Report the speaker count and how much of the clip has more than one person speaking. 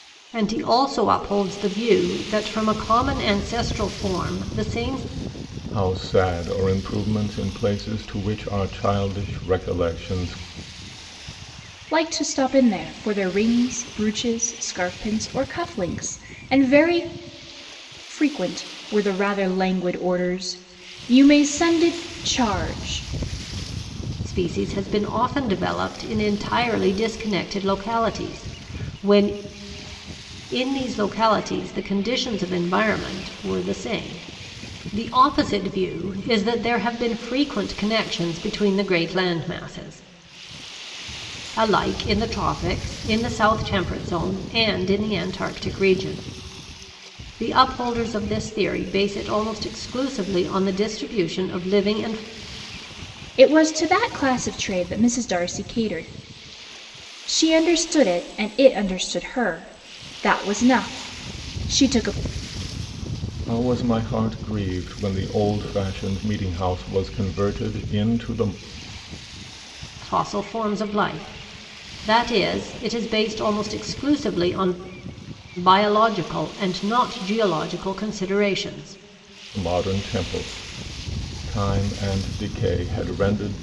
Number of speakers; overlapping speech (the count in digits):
3, no overlap